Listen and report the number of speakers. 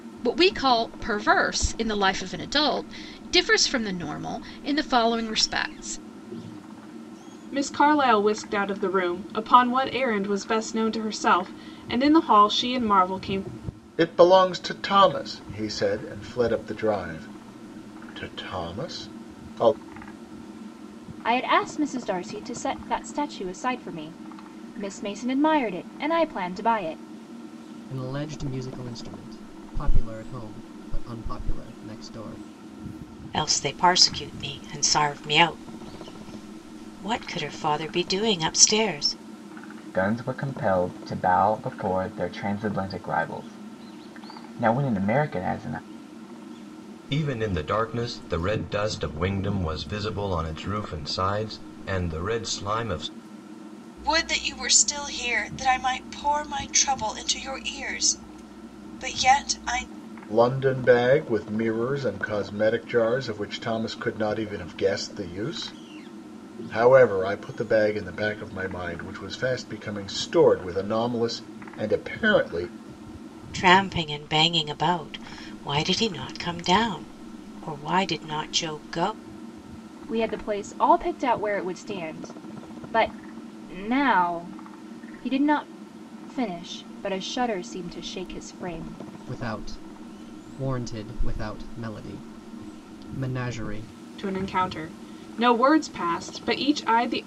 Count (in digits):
9